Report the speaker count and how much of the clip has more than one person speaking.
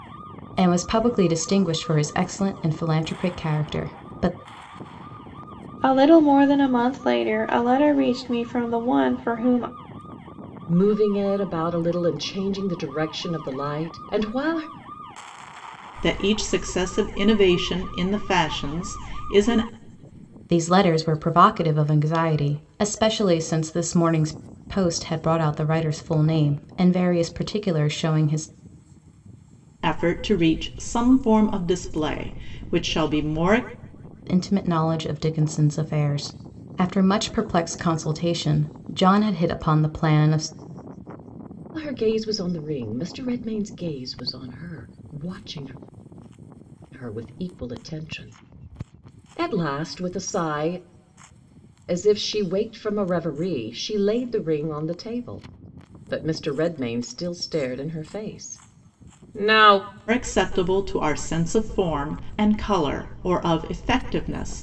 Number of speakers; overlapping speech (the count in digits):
4, no overlap